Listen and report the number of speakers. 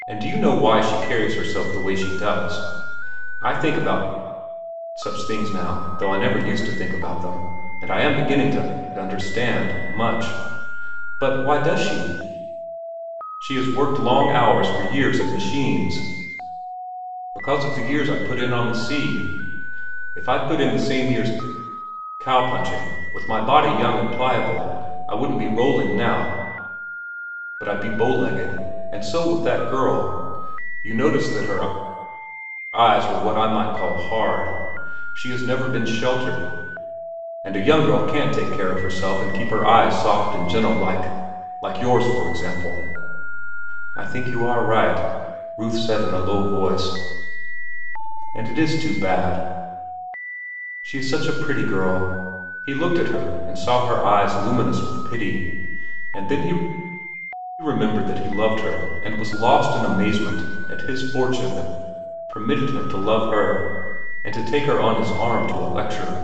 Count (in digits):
1